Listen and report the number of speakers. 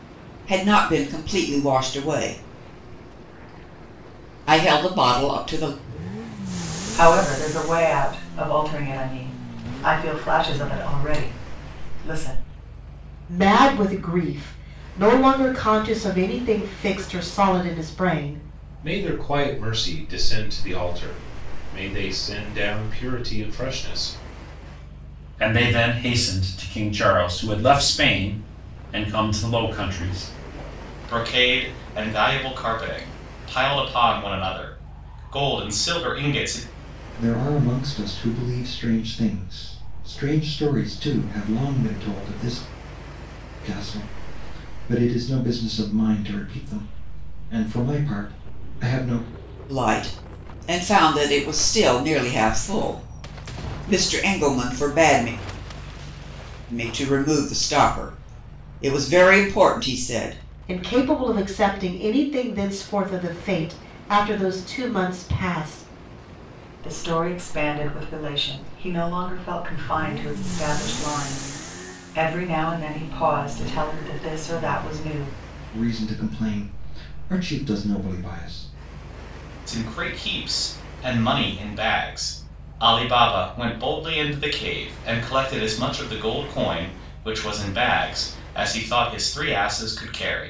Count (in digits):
7